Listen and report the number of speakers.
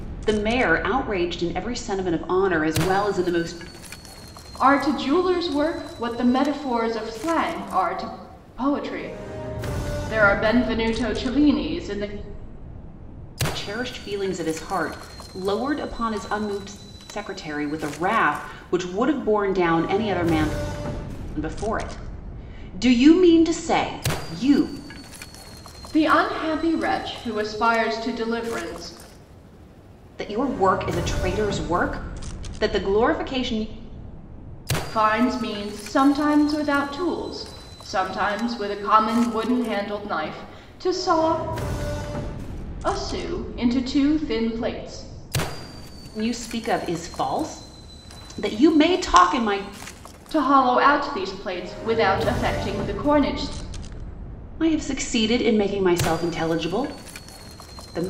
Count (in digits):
2